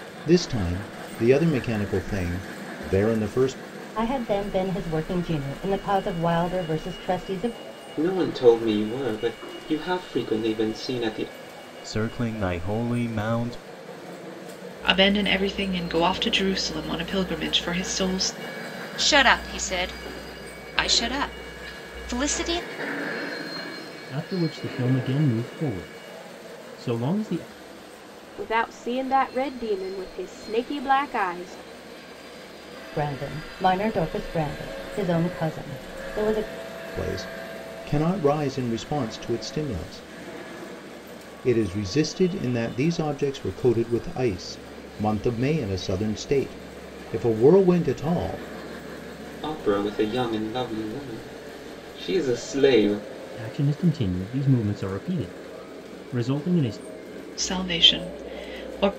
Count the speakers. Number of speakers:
8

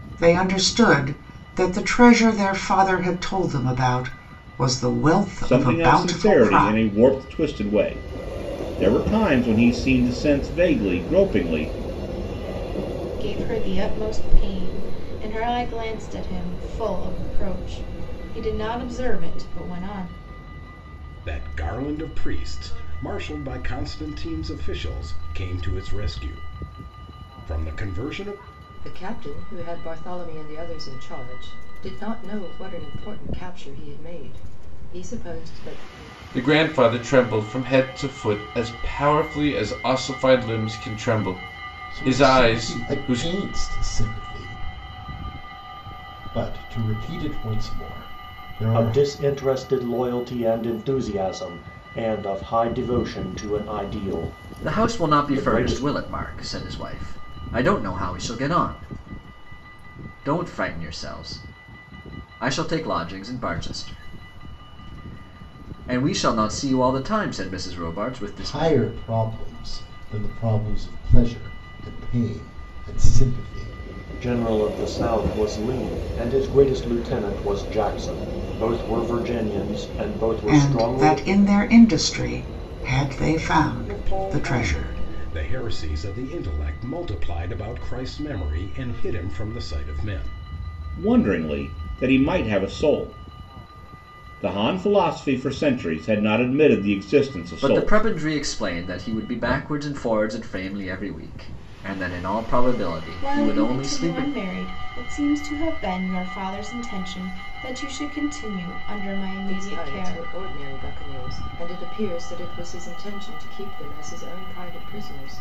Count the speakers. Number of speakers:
9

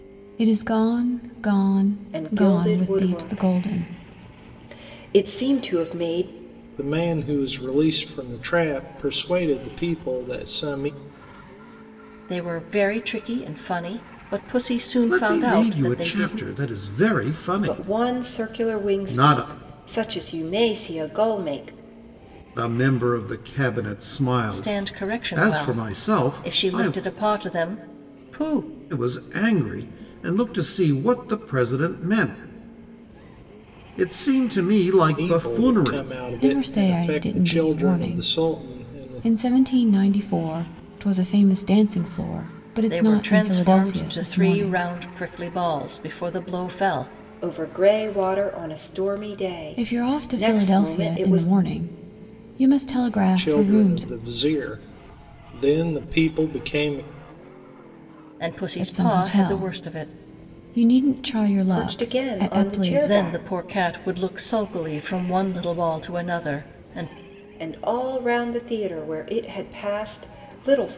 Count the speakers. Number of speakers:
5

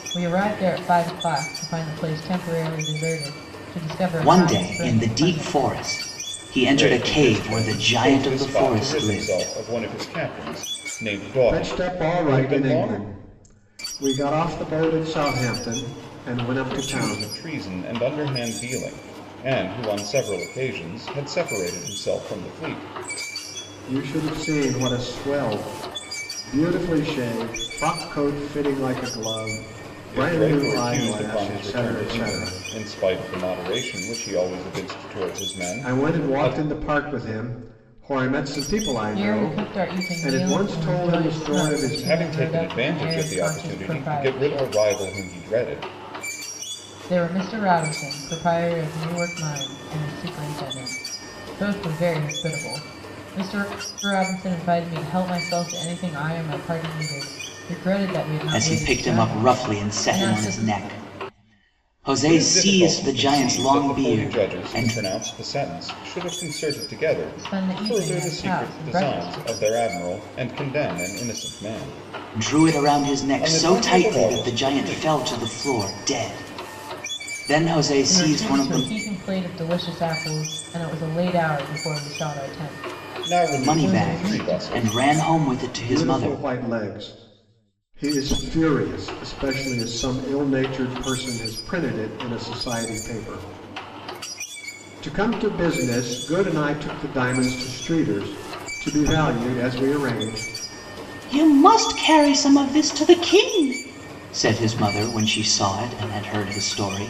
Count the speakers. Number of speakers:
4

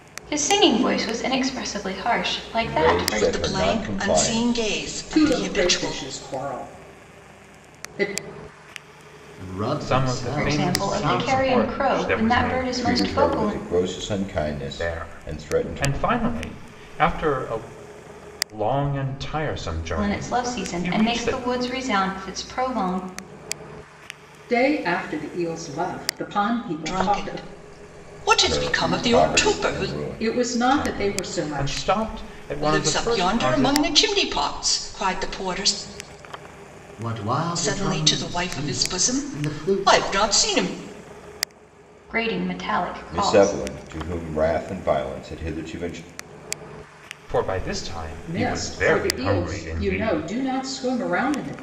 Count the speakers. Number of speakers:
6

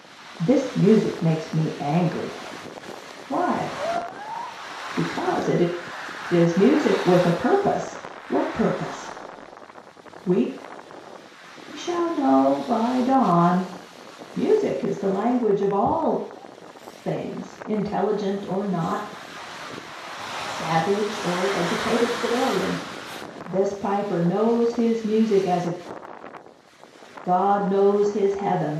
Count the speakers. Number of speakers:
1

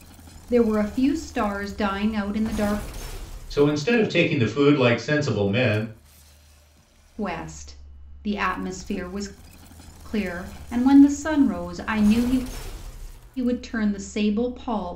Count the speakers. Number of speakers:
2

